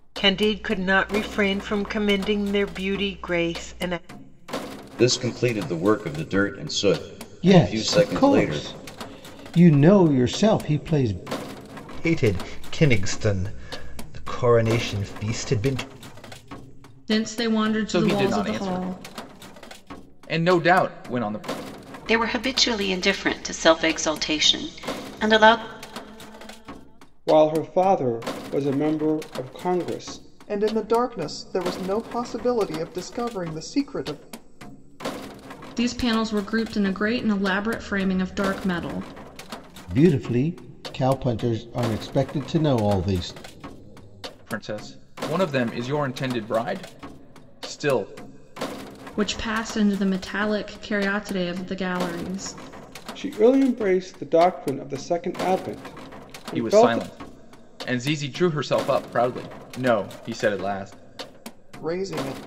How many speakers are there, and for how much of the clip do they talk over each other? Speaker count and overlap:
9, about 5%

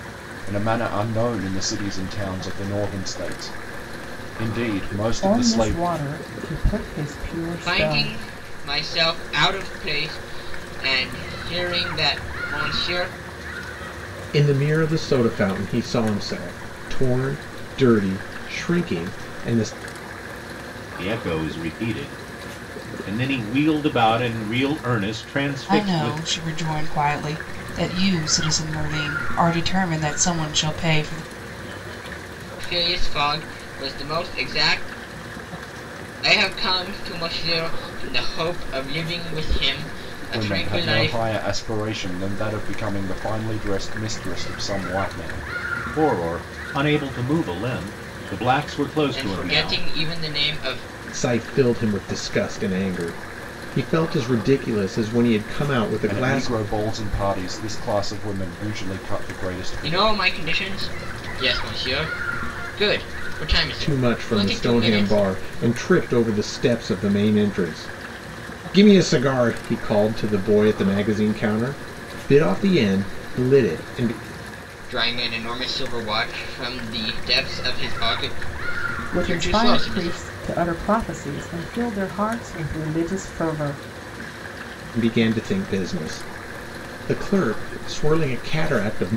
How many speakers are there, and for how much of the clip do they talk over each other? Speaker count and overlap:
6, about 8%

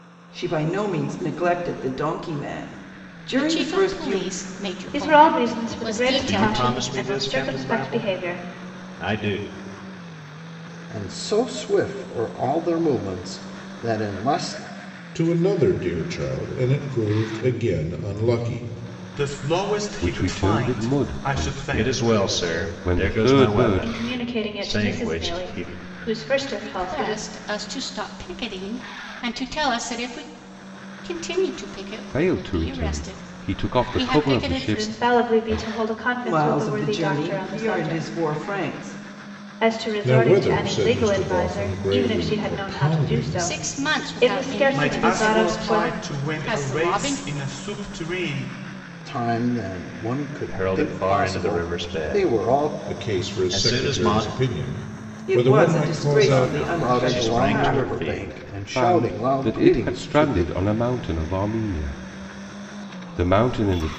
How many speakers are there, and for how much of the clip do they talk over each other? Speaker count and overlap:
8, about 51%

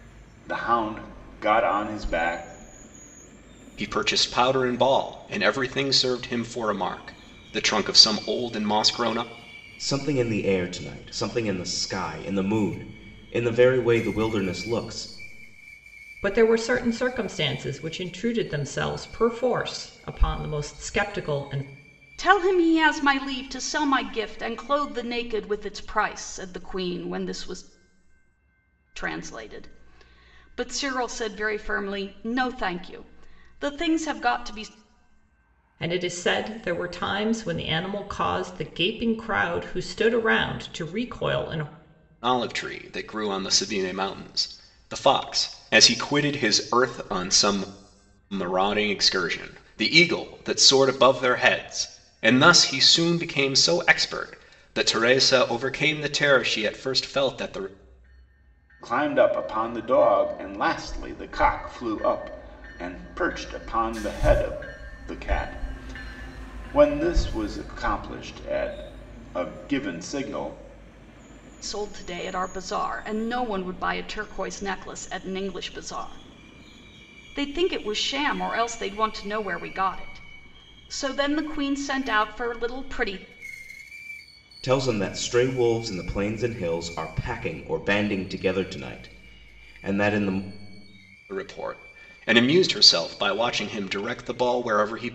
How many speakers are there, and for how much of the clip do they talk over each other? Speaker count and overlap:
5, no overlap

